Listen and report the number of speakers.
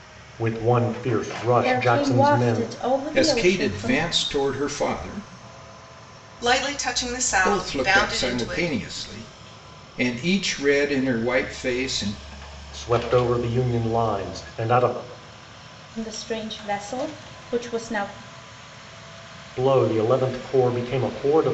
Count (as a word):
four